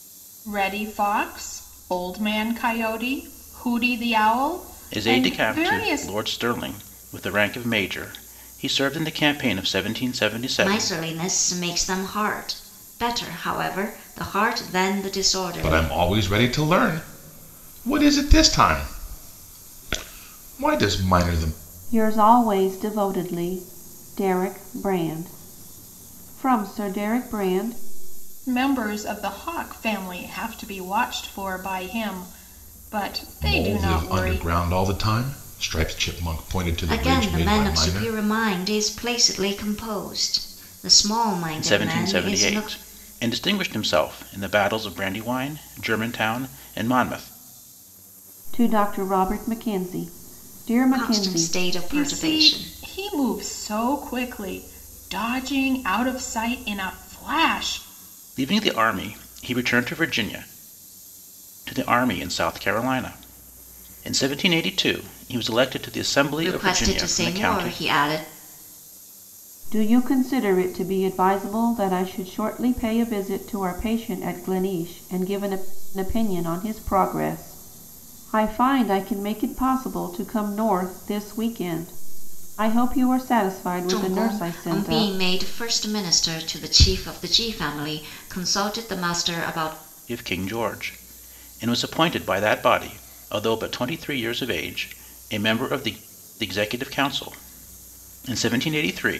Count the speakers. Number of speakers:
5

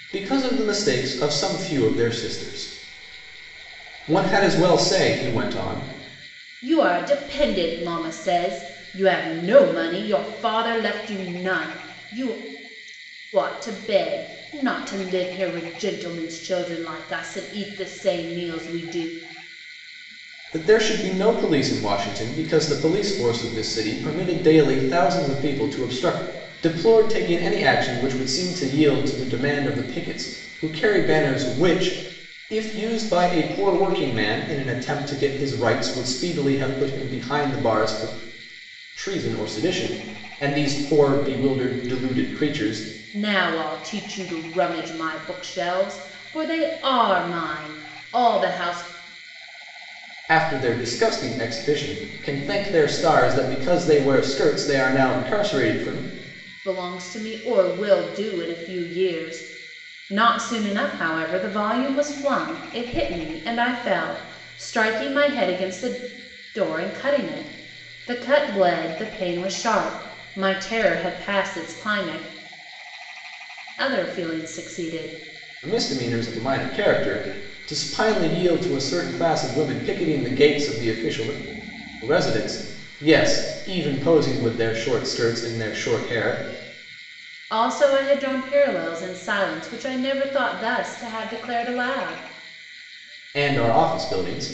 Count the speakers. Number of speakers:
2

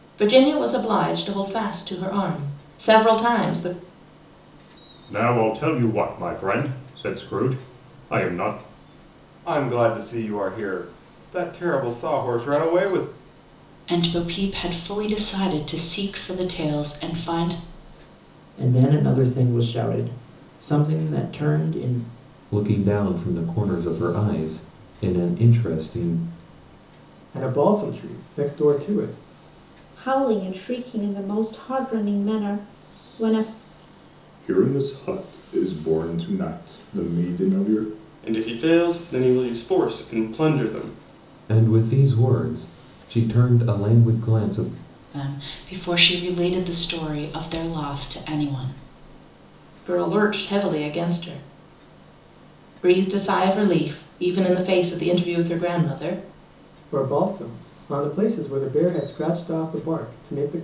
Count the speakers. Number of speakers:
10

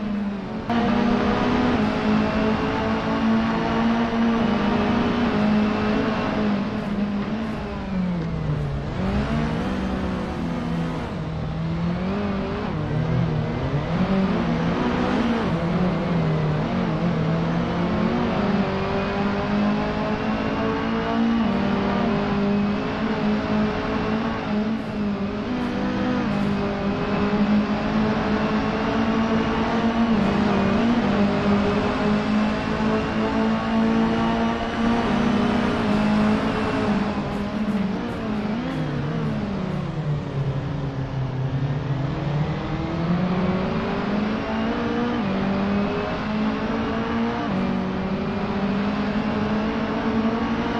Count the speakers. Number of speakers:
0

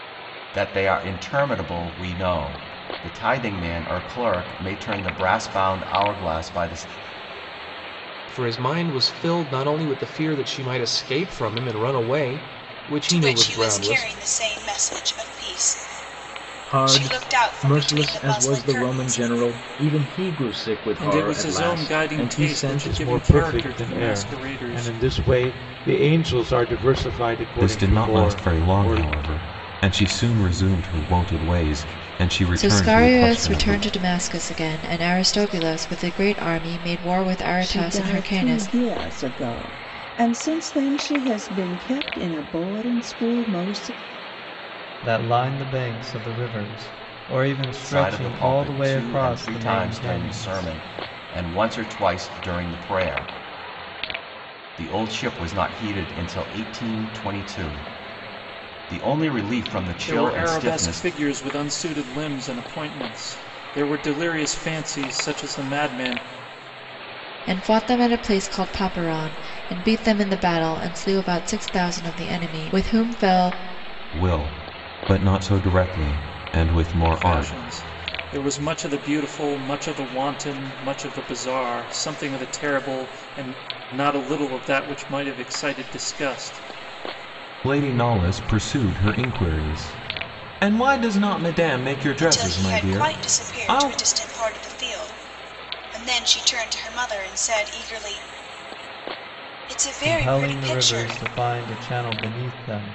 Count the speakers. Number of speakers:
10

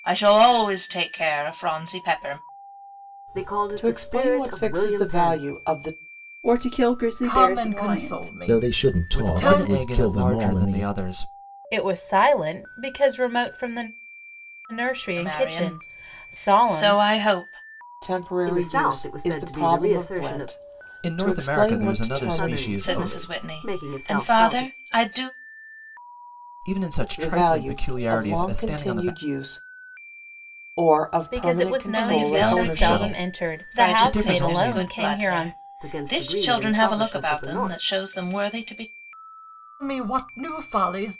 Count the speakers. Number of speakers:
8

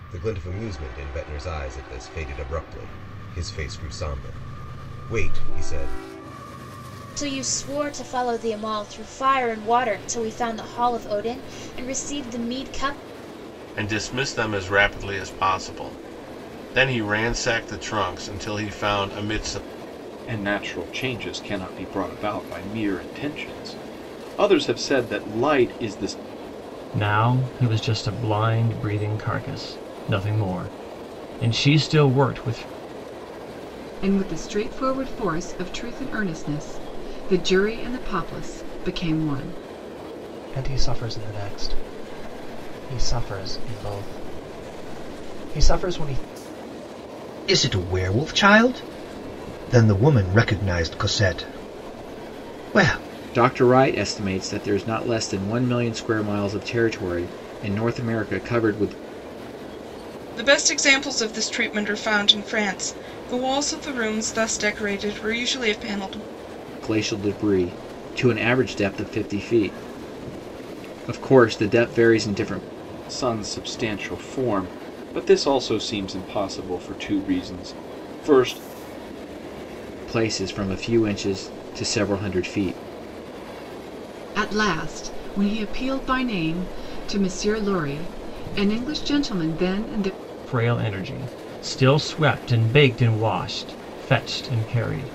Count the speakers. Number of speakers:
10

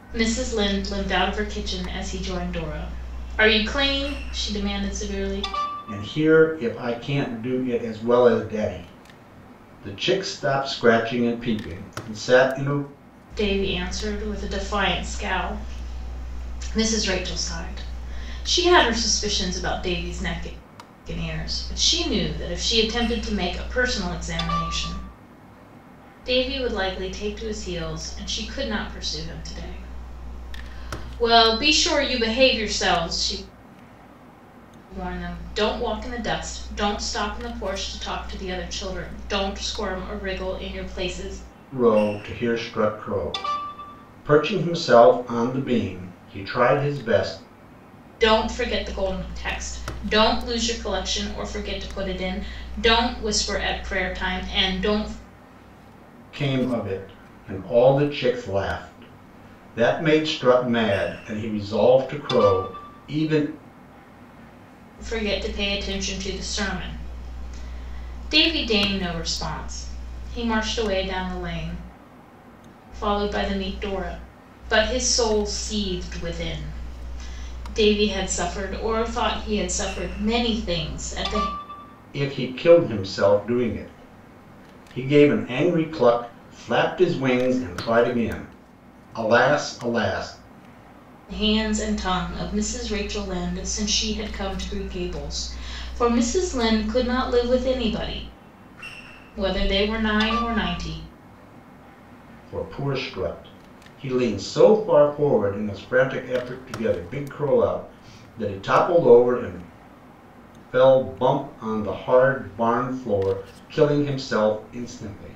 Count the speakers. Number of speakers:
2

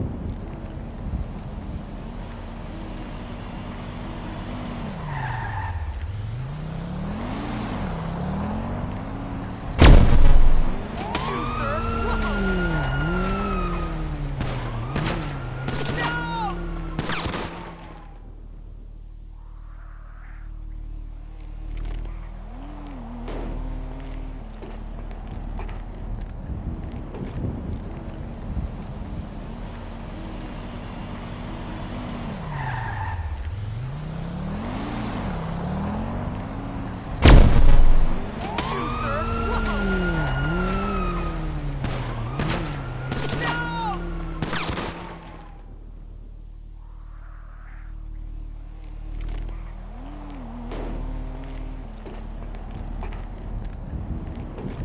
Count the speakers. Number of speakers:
0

